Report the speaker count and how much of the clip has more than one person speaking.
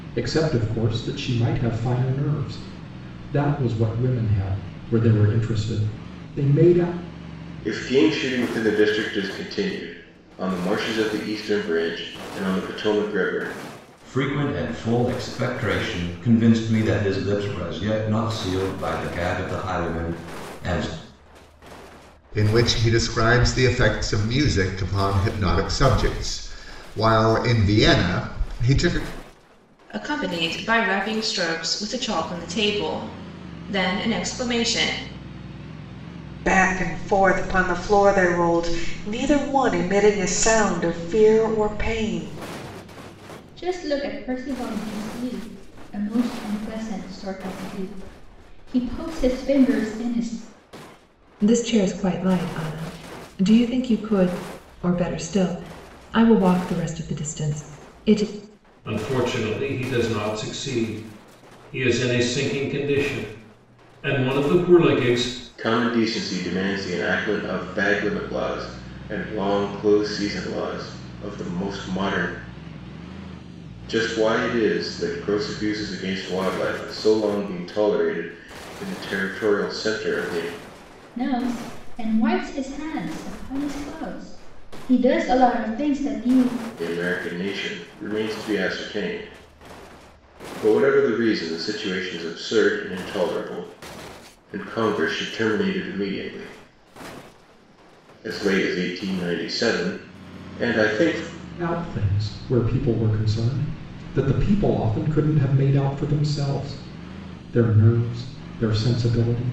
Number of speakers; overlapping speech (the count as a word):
nine, no overlap